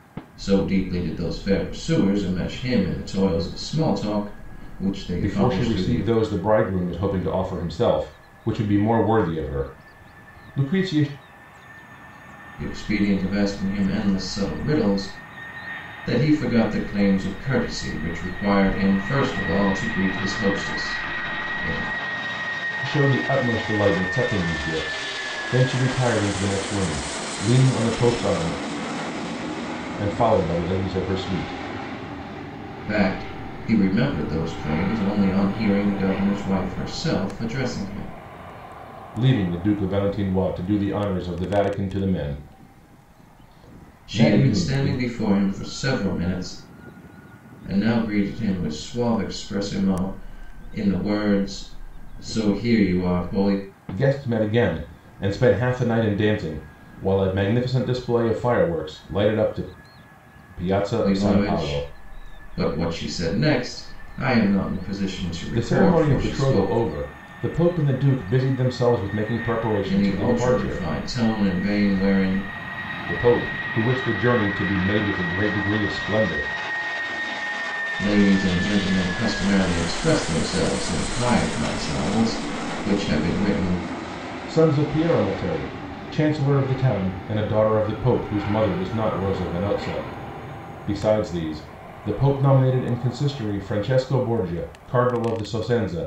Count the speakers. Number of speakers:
2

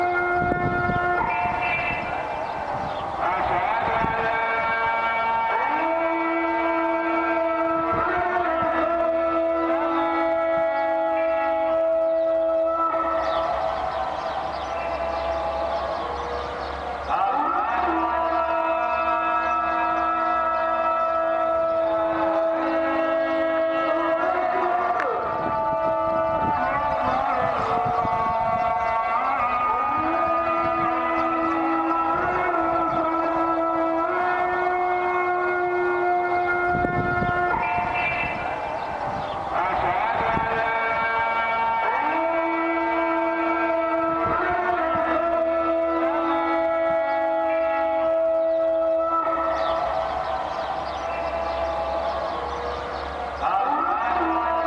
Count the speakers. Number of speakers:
0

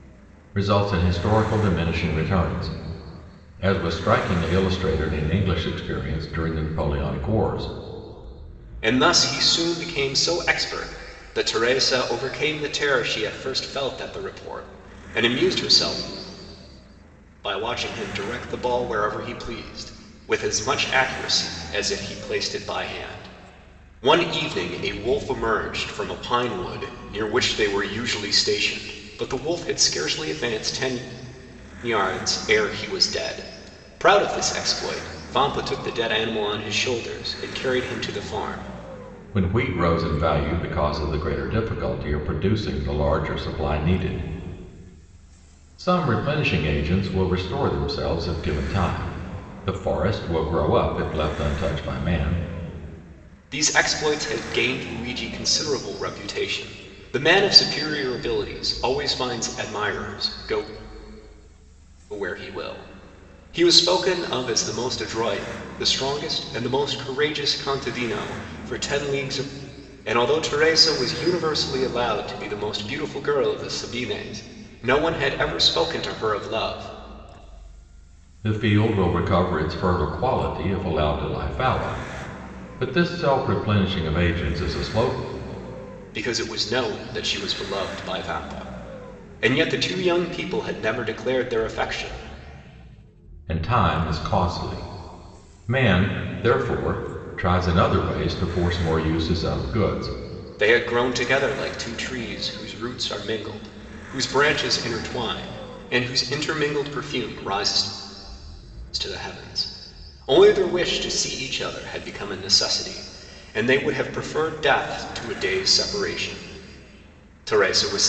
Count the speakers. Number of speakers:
2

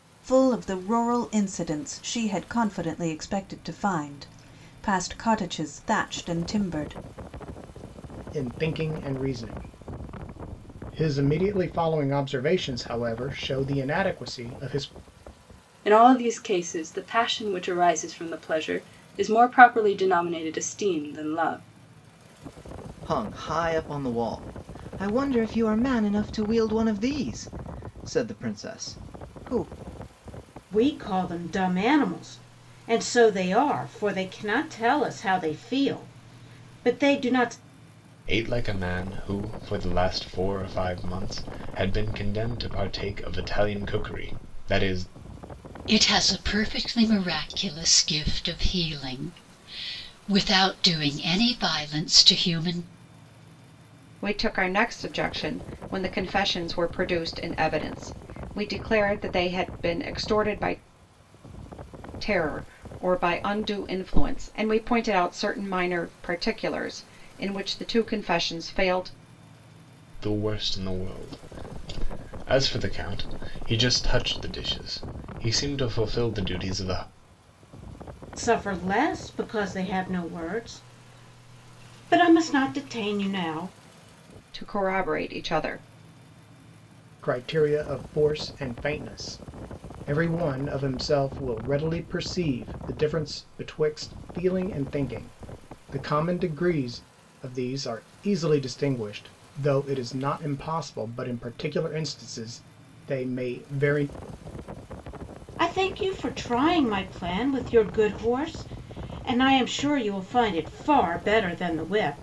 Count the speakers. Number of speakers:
8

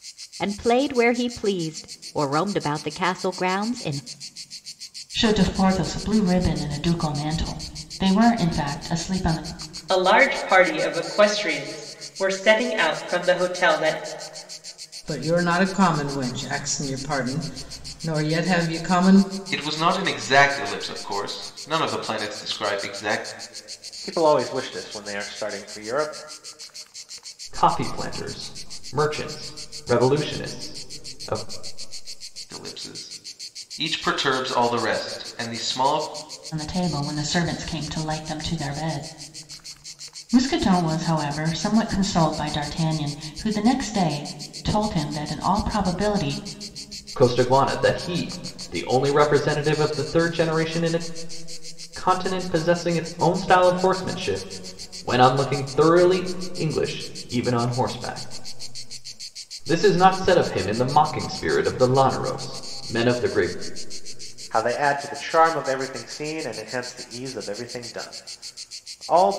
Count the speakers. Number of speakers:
7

